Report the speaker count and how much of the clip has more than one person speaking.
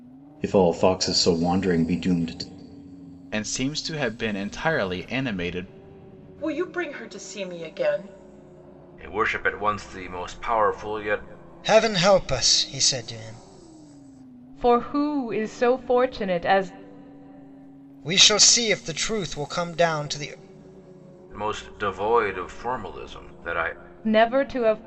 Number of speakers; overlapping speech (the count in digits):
6, no overlap